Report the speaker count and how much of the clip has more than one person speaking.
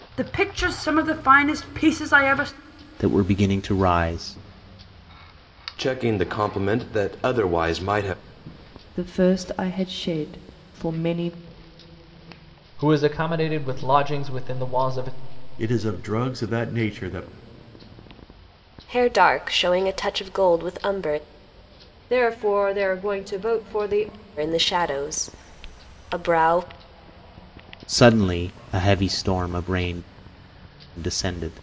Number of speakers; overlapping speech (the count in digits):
8, no overlap